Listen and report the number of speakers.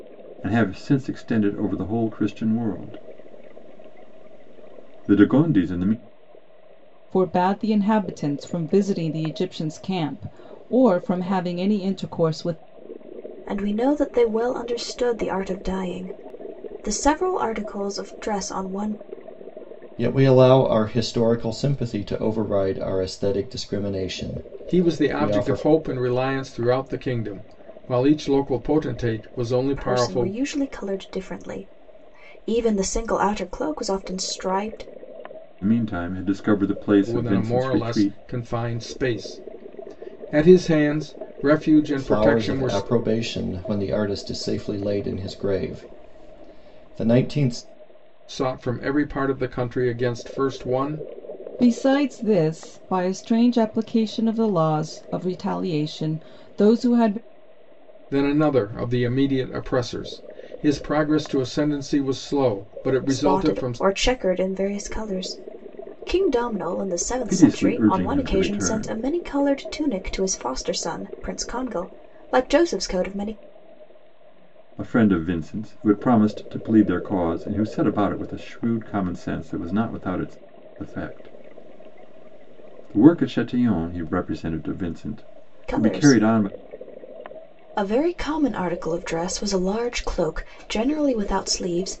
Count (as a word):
five